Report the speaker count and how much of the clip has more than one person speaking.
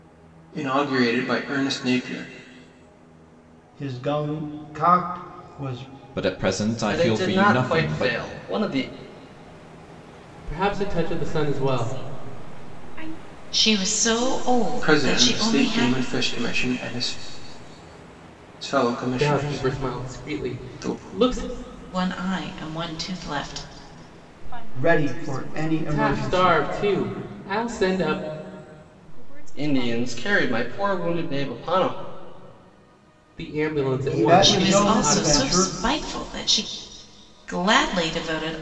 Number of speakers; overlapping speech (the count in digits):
7, about 32%